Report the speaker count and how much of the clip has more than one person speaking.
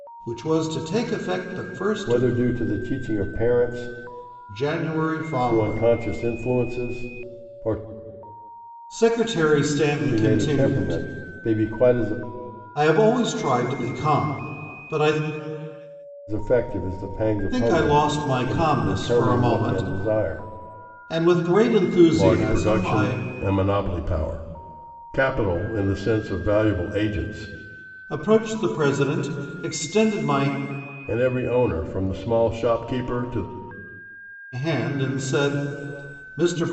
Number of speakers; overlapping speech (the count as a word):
two, about 14%